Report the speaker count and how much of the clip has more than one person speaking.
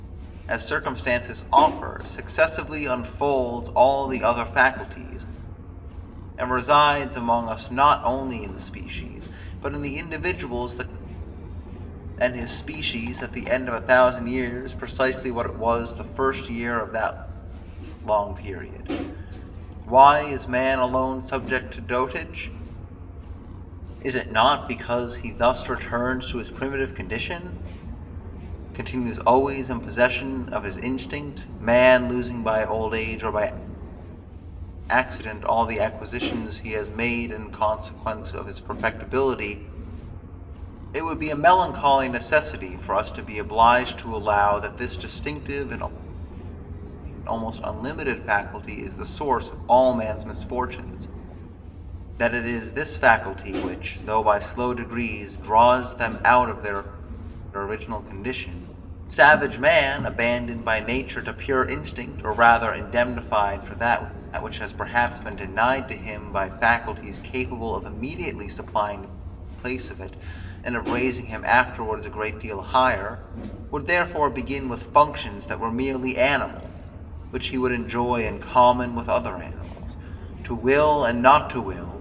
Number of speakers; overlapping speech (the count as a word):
one, no overlap